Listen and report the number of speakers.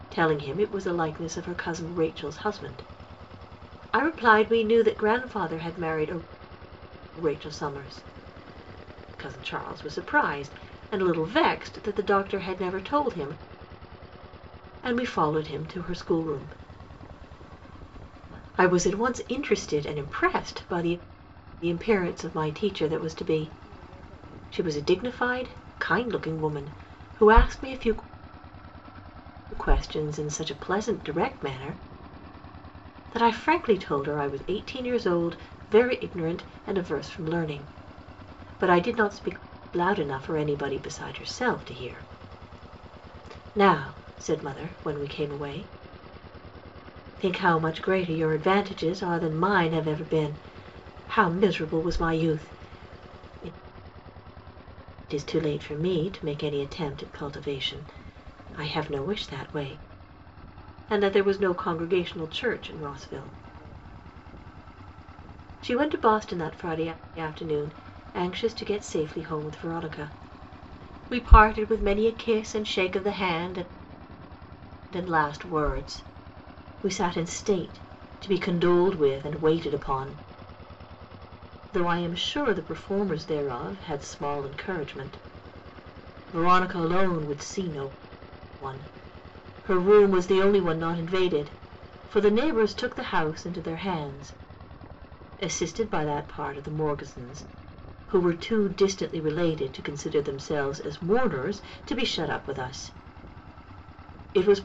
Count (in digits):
1